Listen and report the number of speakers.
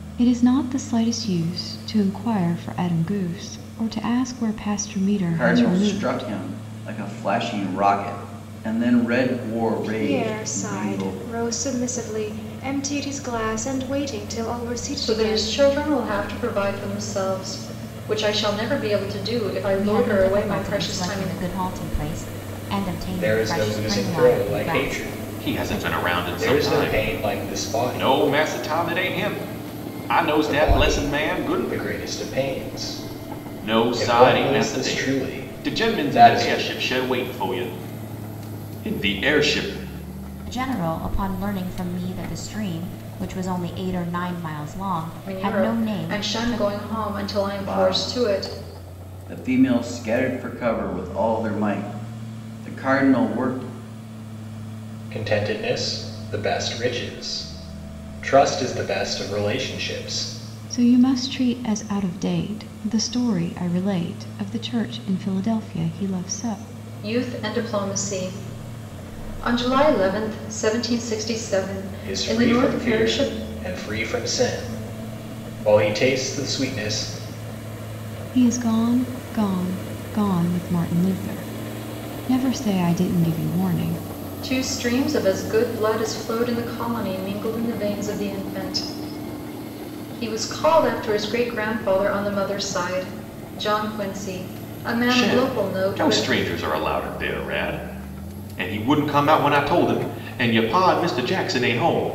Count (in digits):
7